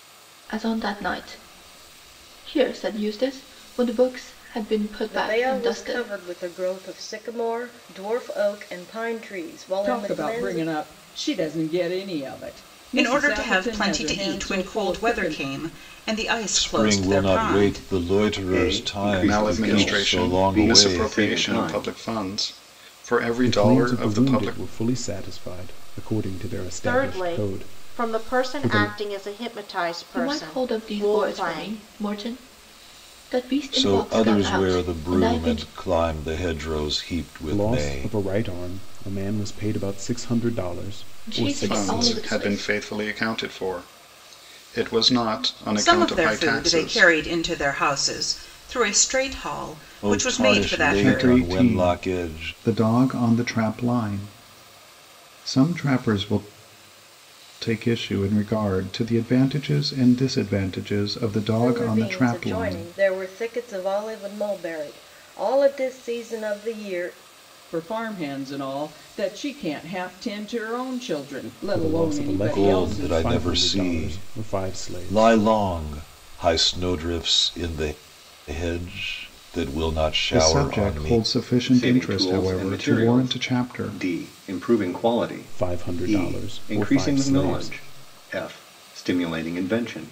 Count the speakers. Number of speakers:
nine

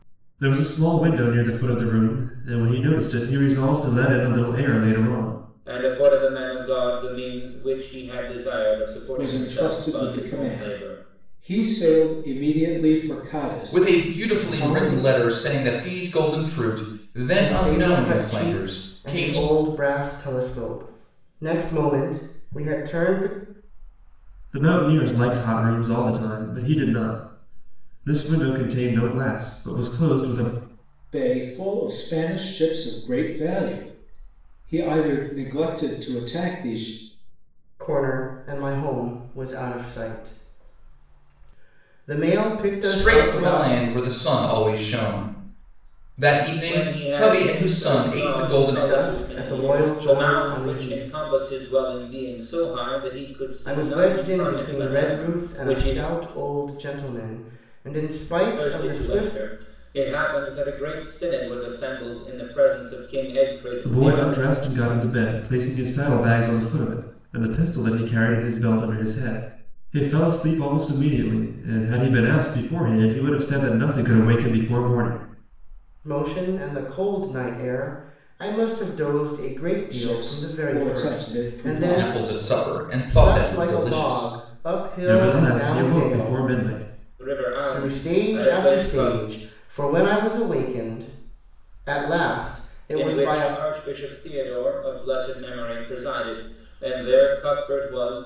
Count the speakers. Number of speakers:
five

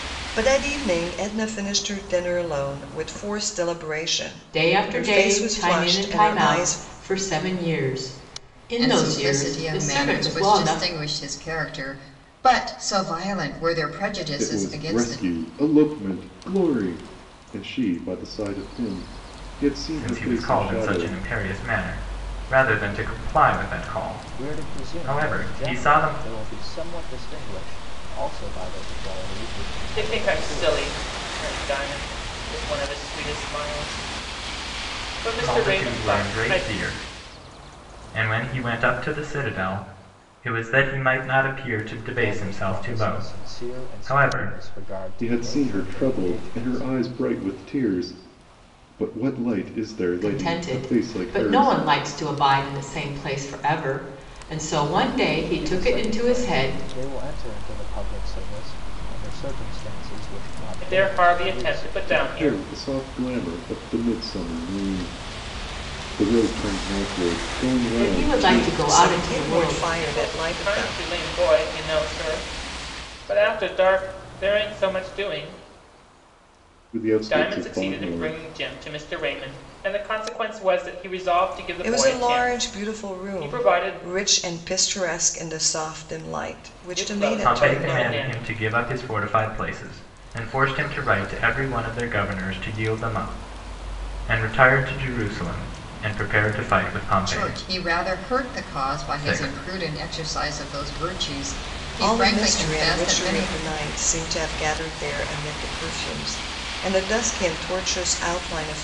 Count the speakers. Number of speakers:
seven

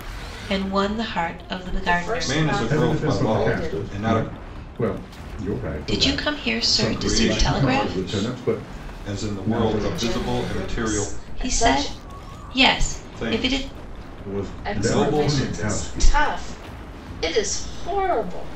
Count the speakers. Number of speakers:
four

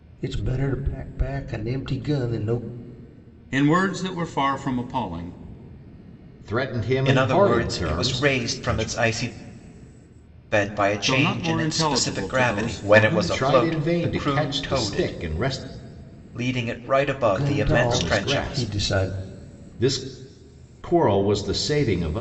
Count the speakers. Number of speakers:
four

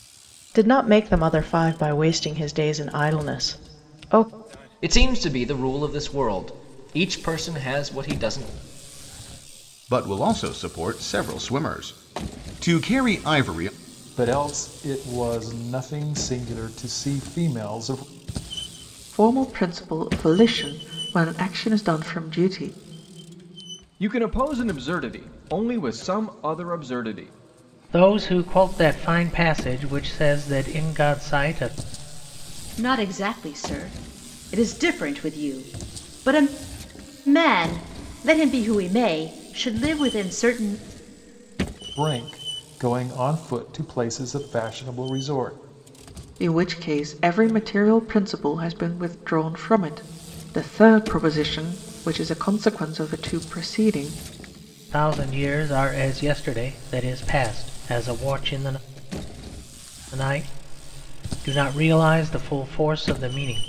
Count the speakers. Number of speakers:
eight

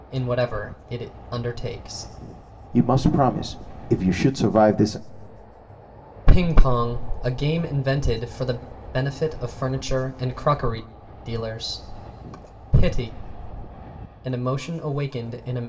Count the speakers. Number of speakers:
two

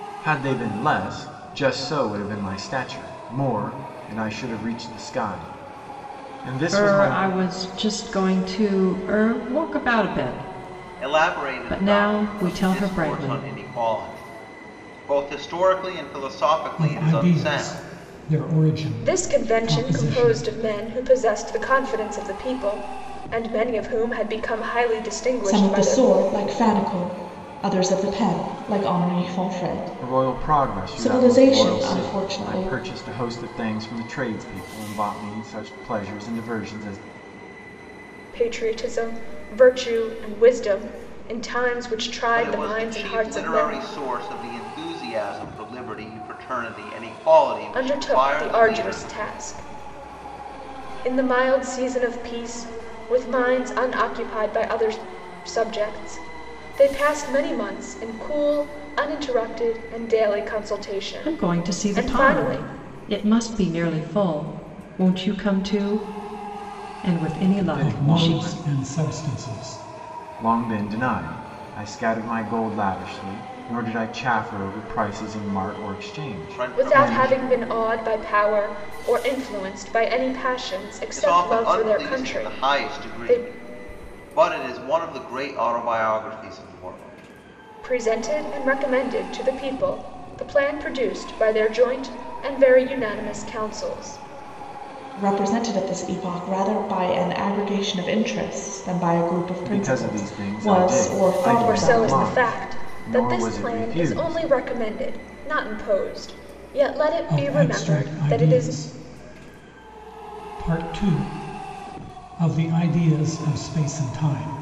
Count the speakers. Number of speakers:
six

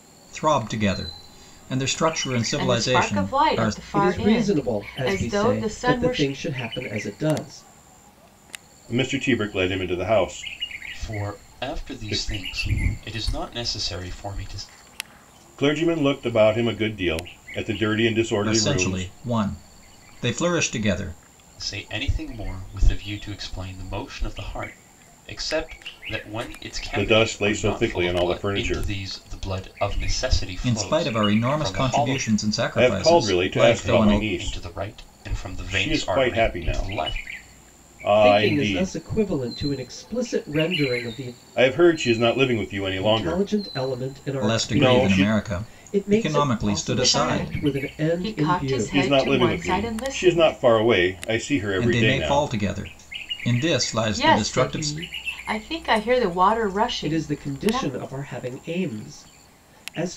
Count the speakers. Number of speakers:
five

